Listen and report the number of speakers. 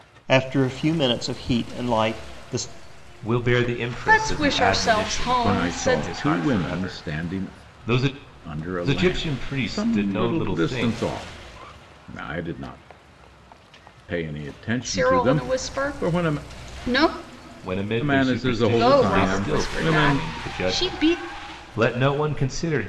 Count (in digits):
4